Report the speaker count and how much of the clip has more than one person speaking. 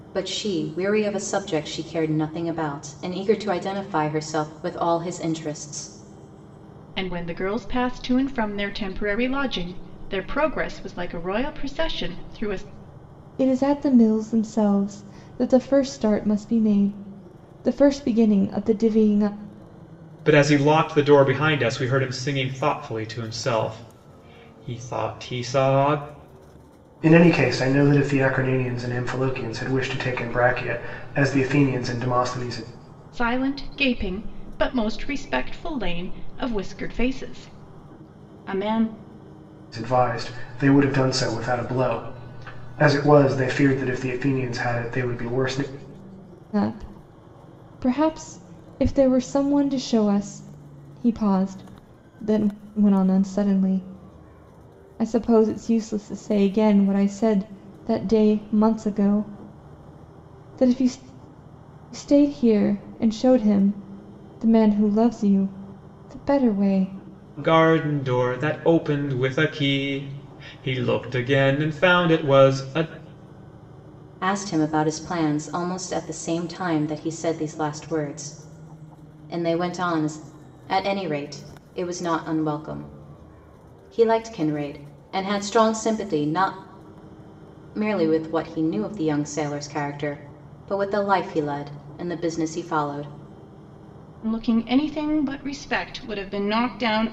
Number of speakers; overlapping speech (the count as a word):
five, no overlap